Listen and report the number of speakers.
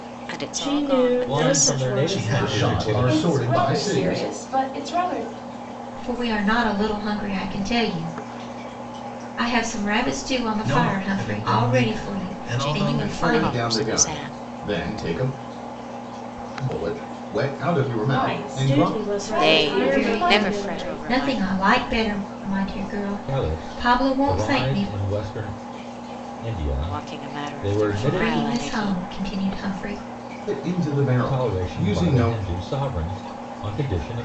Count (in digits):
7